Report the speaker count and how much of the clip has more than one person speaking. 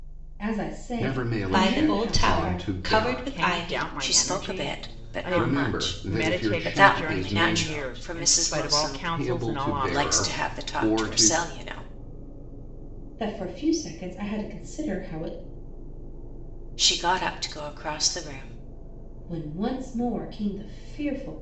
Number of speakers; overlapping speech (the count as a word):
five, about 47%